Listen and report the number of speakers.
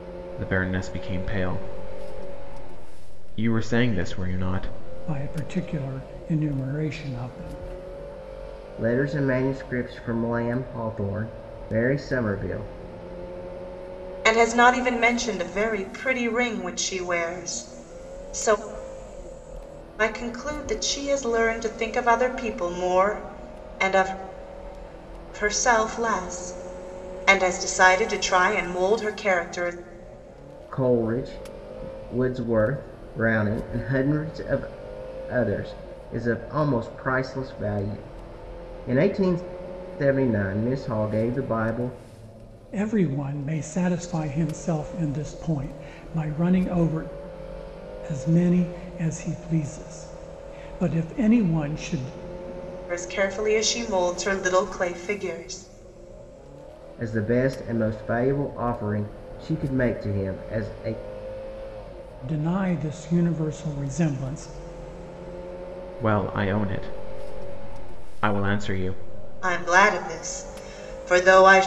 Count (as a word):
four